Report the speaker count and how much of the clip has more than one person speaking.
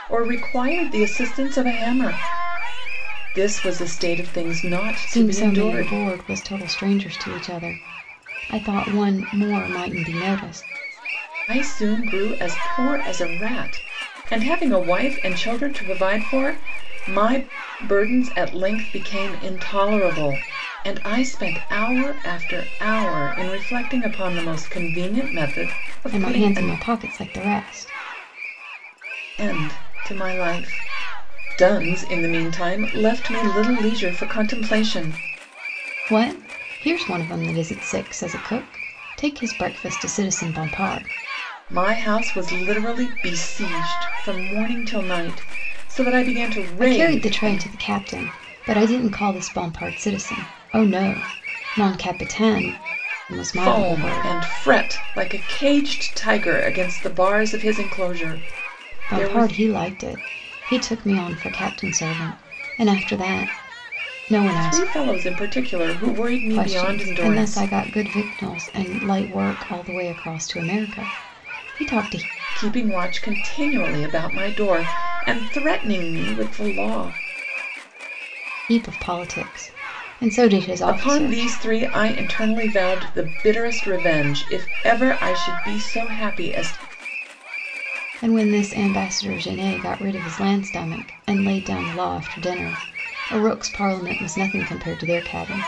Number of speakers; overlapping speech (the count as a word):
two, about 6%